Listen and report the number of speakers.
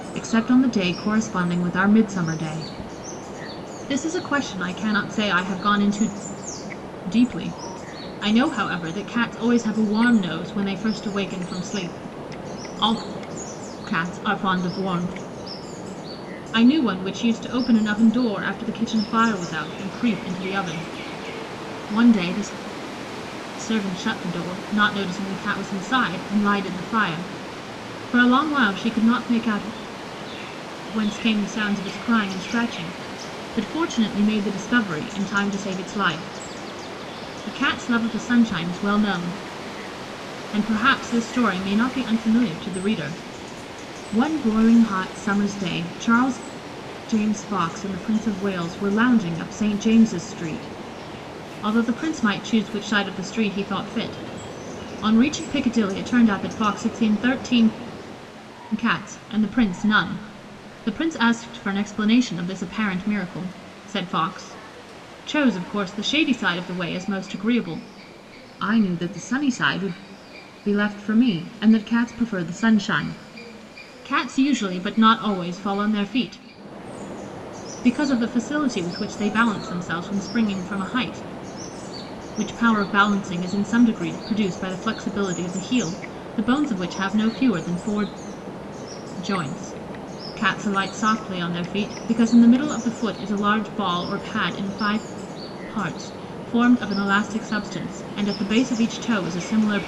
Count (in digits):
1